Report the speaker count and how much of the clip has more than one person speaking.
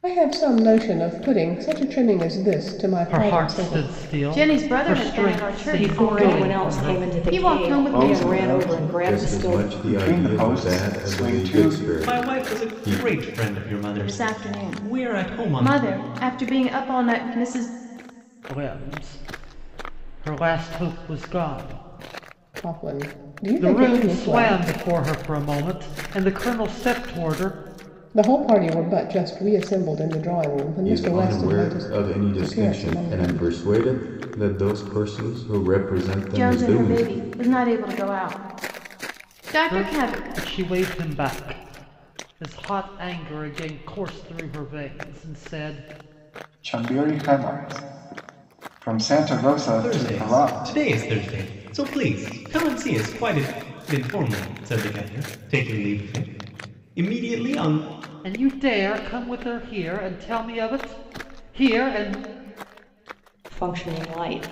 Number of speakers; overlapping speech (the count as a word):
seven, about 26%